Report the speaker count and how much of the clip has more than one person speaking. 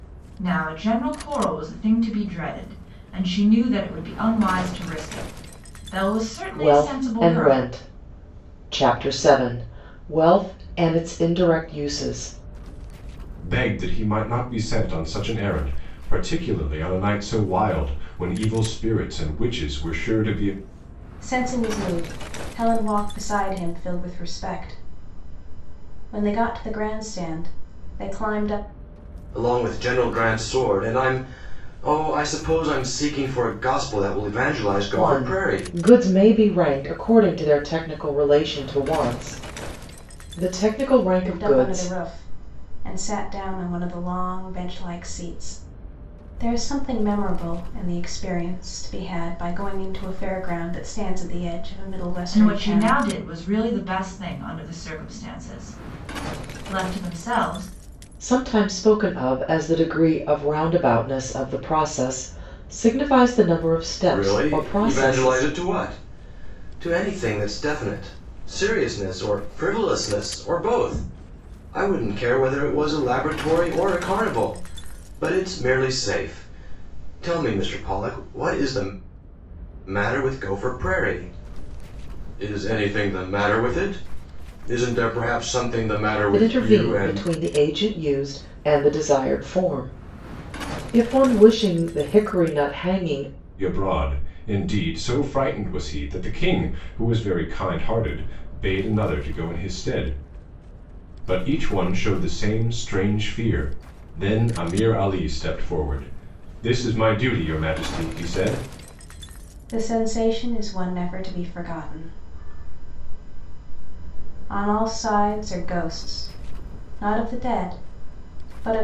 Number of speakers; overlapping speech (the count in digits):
5, about 5%